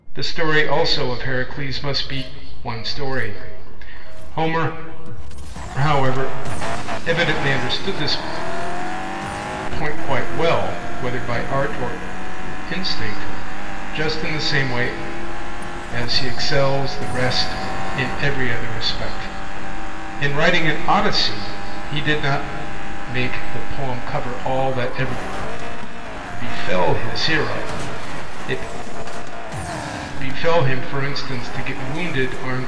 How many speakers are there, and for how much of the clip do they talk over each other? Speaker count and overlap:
one, no overlap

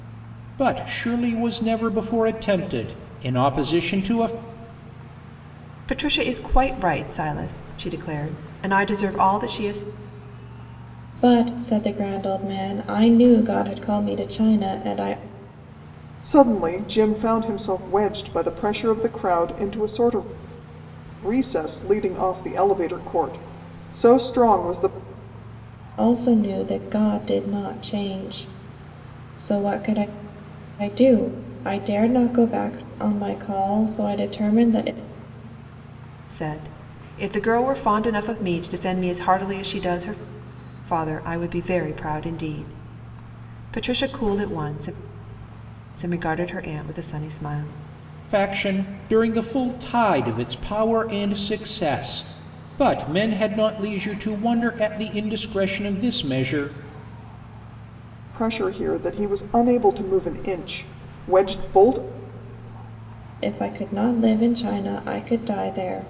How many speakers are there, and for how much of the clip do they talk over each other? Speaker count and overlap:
four, no overlap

